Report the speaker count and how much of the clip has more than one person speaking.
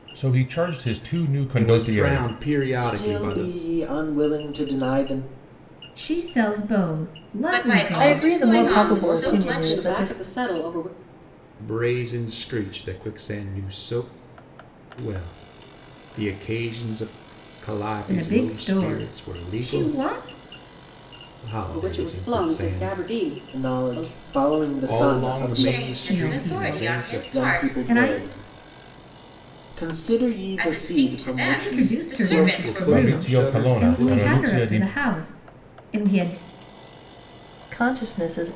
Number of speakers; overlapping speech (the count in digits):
7, about 41%